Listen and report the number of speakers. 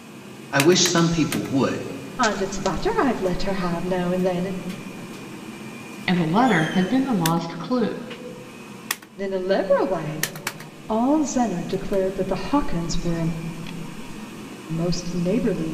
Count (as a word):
three